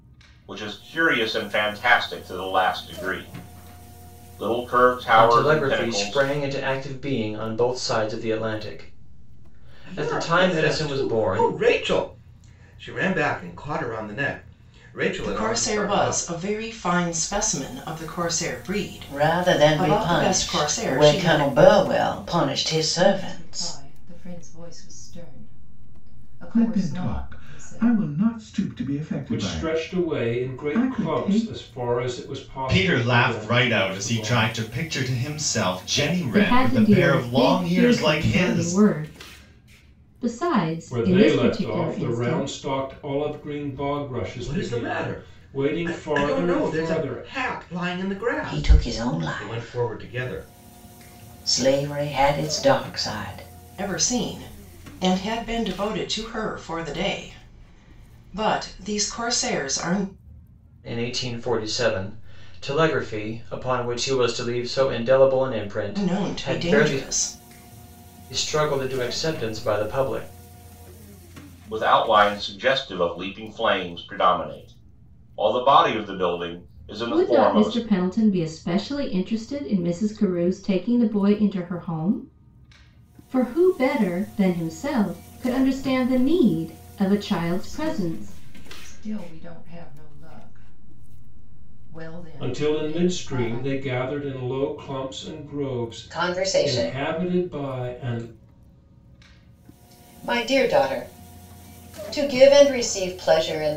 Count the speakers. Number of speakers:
10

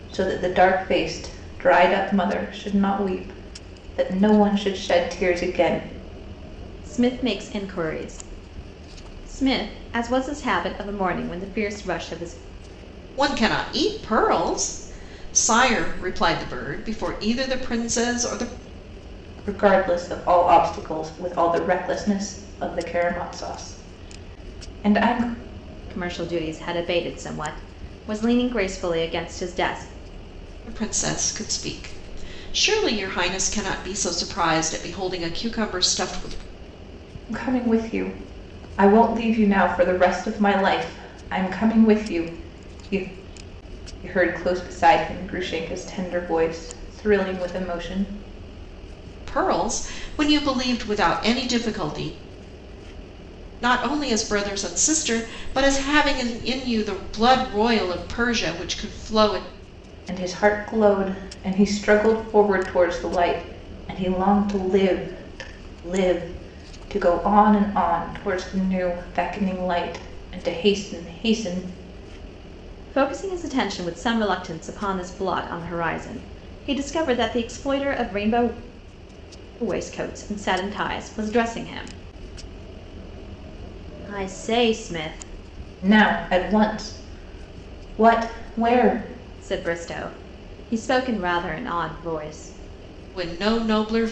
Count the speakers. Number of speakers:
3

